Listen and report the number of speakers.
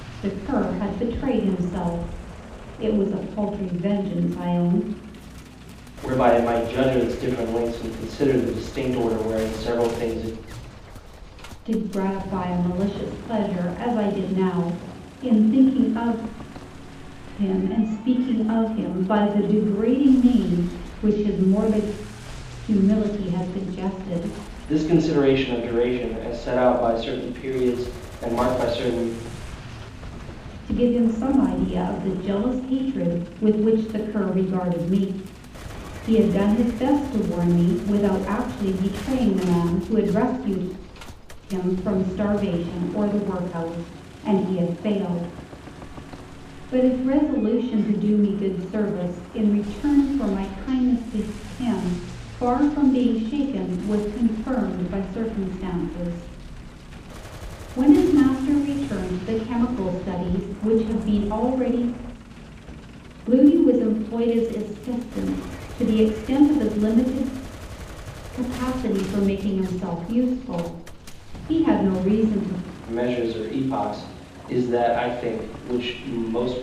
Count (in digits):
2